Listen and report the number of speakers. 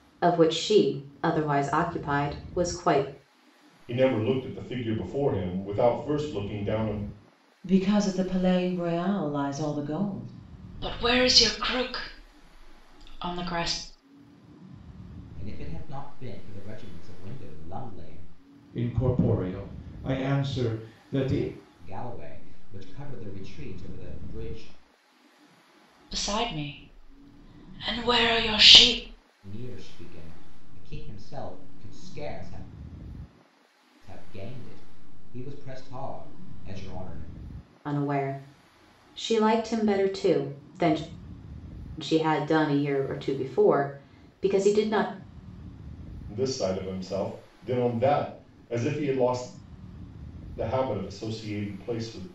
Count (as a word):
six